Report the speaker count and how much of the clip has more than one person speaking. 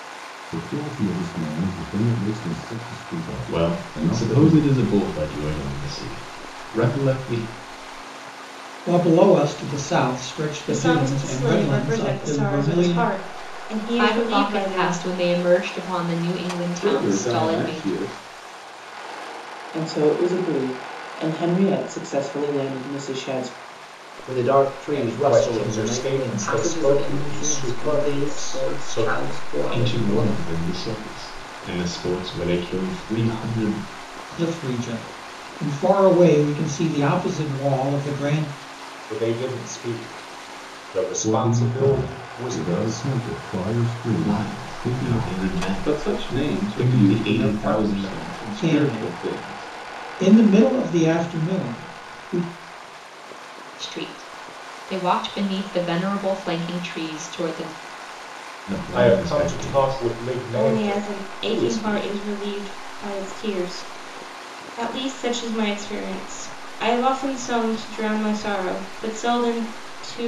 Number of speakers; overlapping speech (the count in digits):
10, about 29%